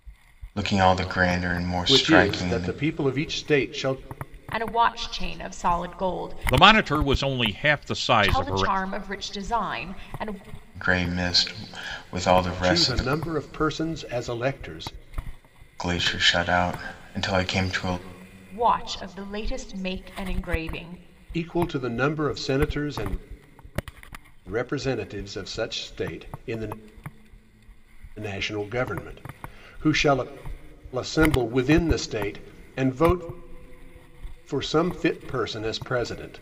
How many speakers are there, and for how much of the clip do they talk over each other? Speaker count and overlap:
four, about 7%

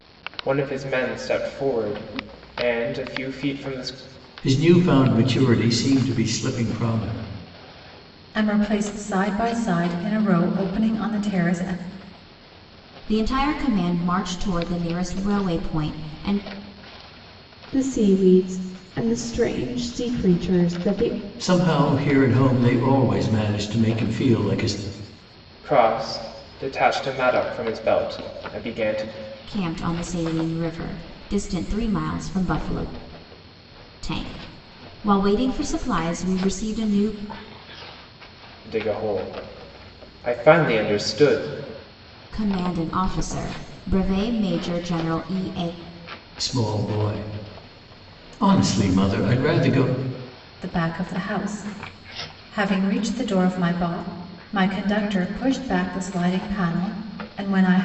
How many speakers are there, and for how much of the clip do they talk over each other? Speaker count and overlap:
five, no overlap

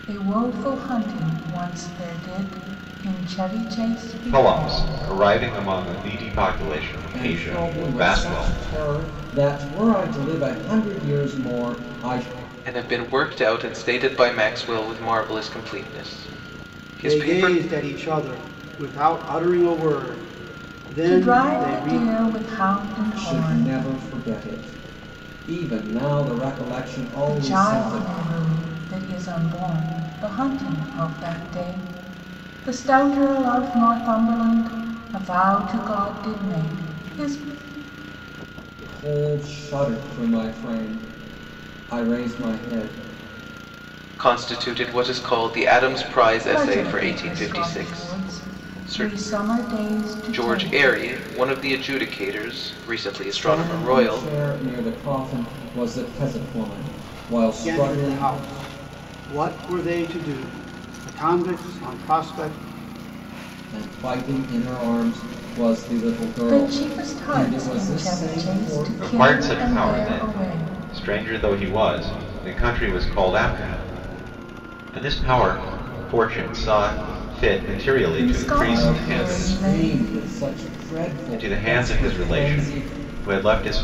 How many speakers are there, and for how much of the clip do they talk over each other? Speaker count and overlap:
five, about 22%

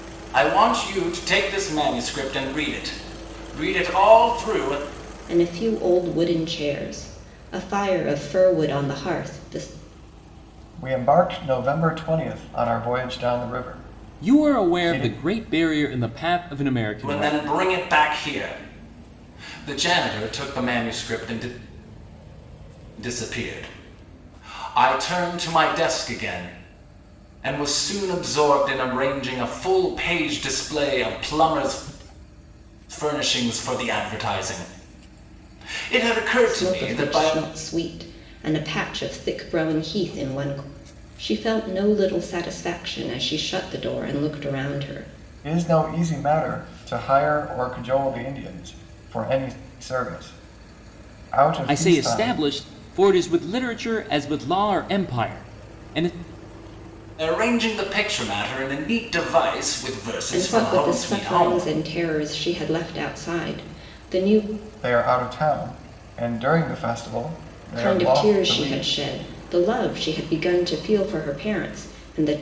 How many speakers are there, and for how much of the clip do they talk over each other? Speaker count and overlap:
four, about 8%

